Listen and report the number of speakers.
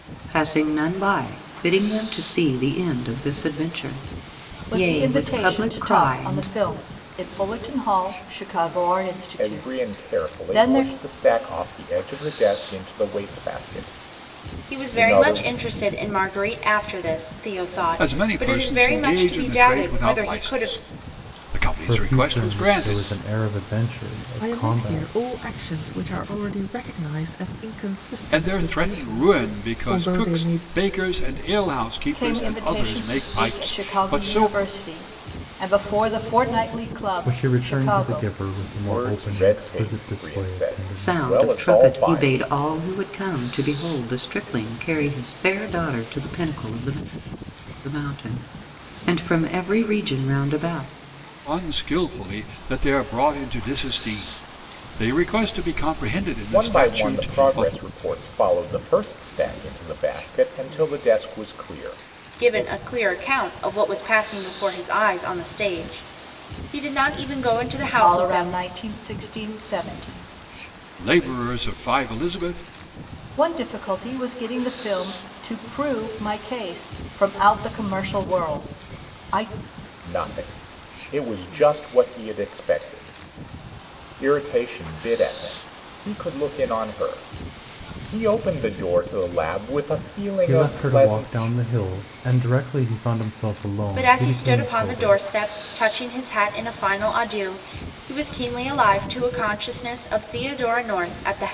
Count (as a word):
seven